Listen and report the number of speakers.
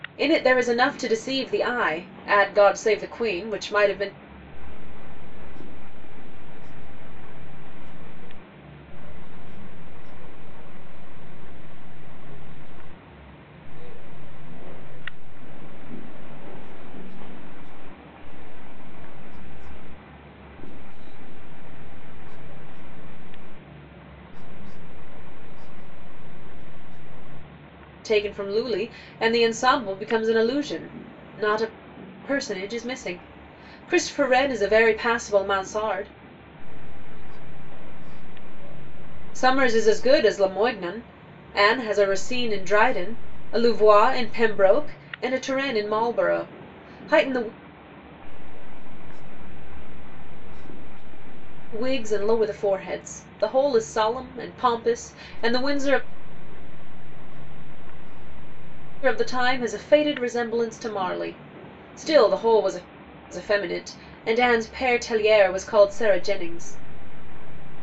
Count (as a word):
two